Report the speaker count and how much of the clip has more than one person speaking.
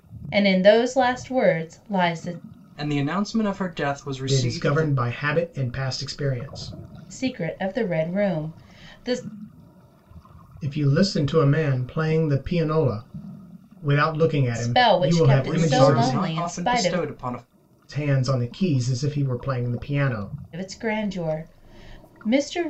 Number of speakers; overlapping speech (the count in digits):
3, about 14%